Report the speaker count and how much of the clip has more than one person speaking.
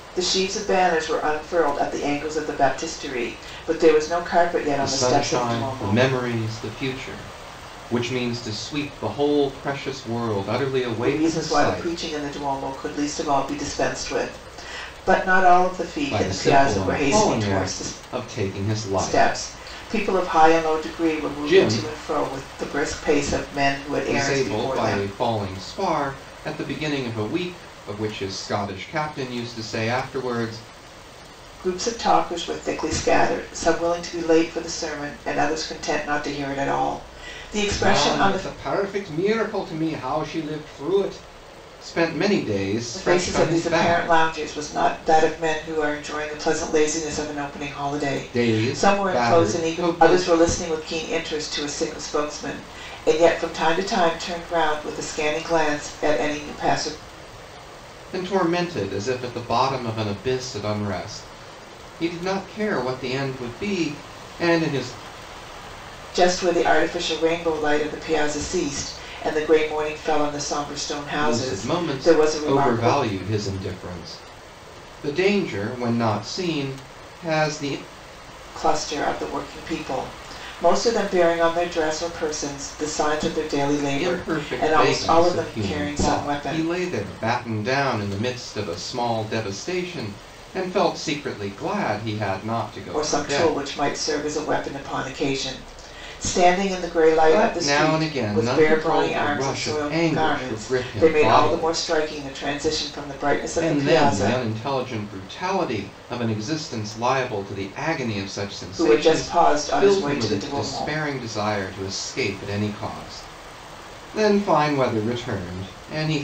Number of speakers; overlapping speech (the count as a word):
two, about 21%